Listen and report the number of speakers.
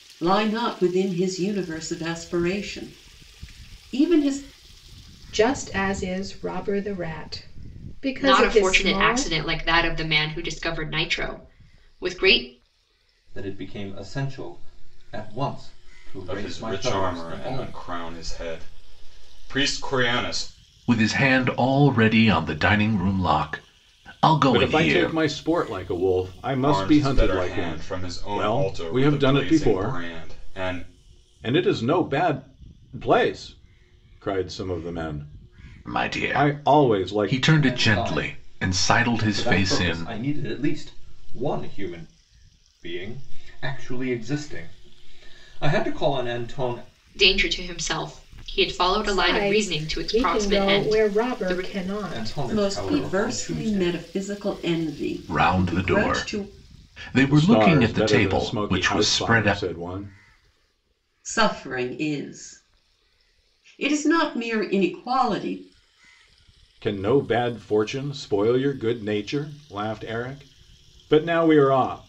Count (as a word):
seven